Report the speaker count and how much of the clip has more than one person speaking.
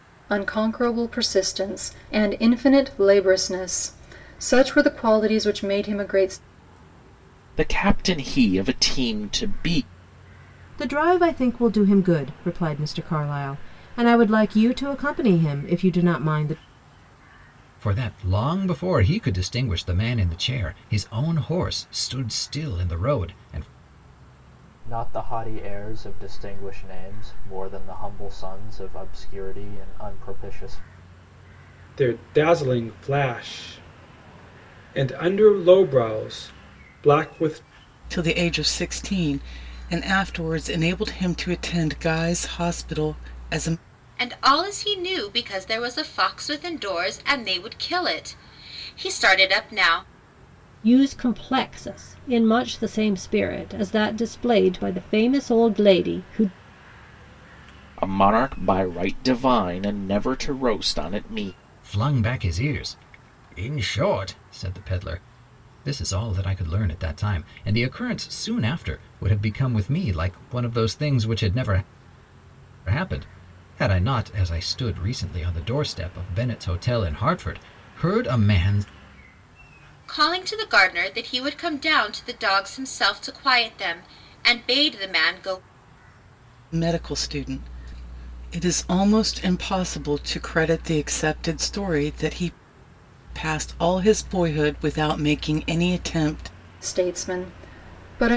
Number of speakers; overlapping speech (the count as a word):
nine, no overlap